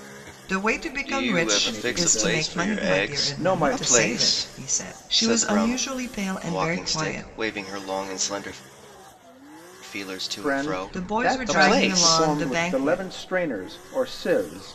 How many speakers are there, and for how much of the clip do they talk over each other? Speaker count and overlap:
three, about 58%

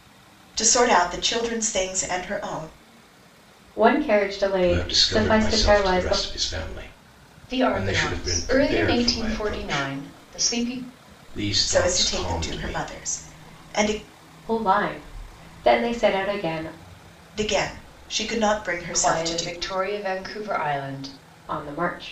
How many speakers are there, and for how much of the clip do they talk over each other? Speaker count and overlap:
four, about 26%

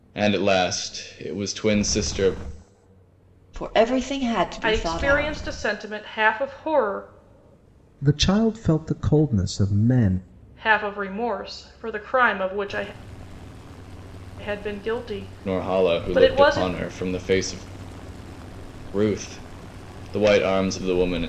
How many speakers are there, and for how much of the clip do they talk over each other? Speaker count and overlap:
four, about 10%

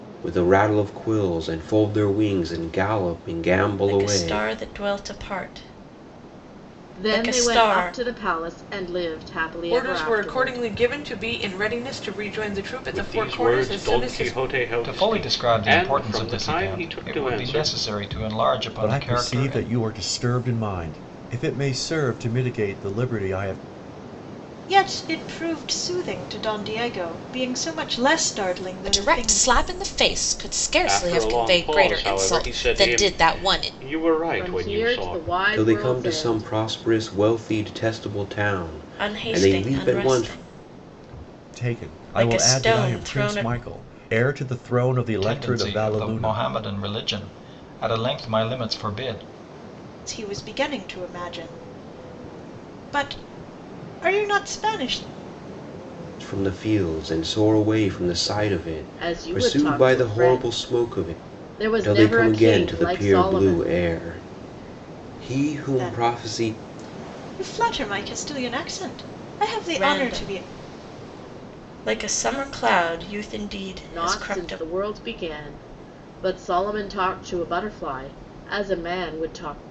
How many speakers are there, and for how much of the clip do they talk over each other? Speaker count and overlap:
nine, about 31%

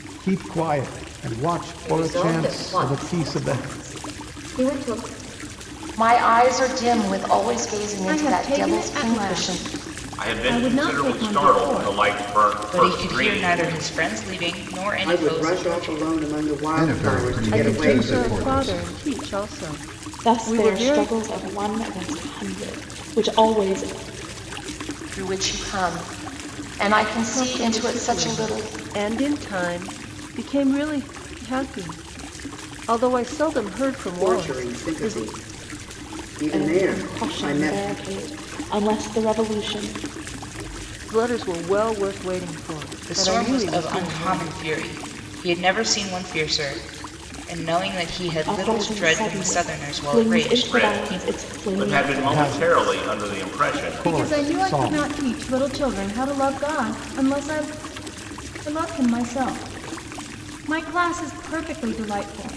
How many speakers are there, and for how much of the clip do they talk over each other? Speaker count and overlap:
ten, about 36%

